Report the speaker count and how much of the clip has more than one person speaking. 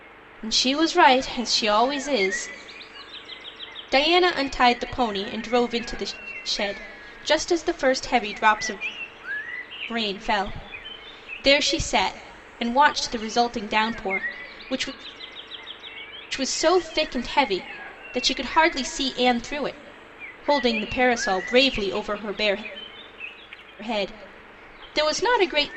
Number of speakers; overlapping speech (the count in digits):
1, no overlap